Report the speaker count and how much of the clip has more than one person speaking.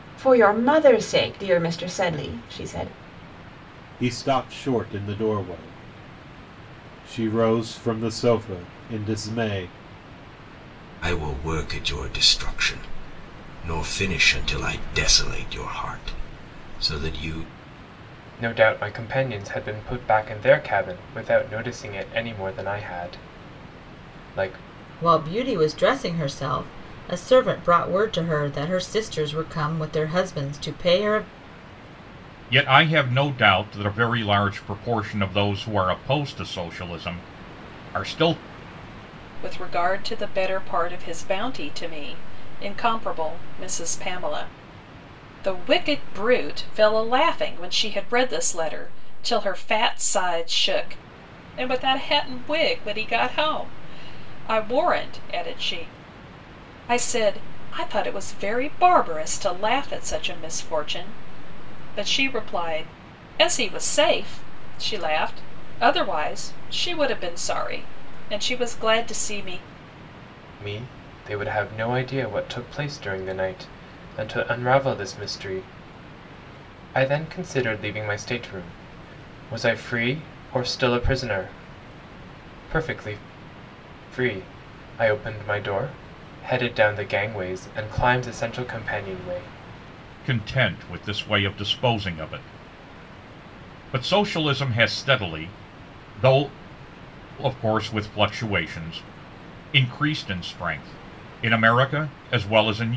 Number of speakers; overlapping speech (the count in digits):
7, no overlap